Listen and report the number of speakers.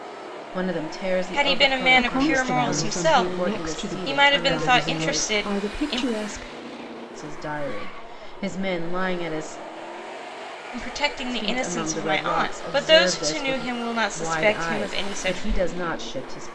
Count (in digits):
3